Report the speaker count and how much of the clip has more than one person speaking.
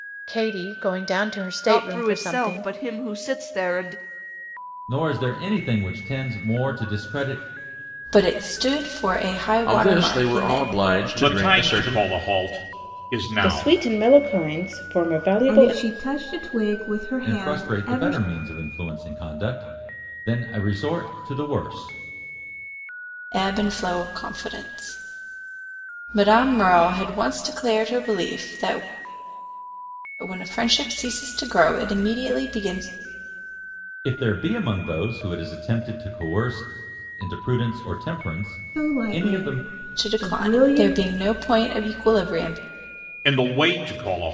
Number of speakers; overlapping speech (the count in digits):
8, about 15%